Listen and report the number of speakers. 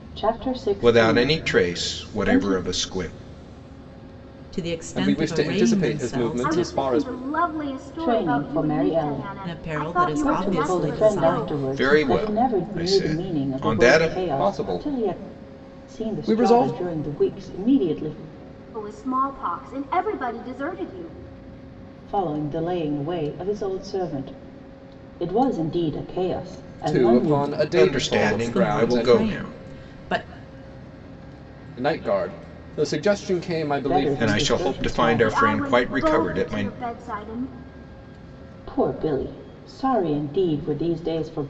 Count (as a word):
five